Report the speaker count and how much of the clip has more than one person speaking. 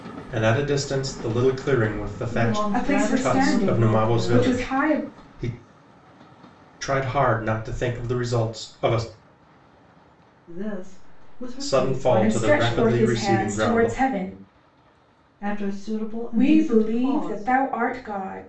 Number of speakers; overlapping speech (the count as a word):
three, about 34%